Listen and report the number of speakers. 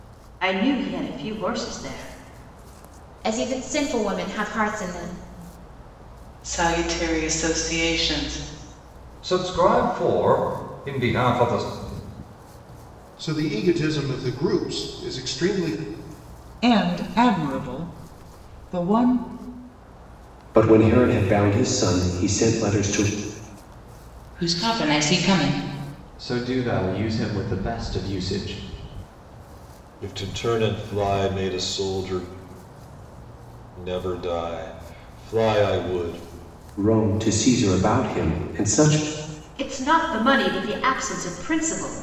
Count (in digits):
10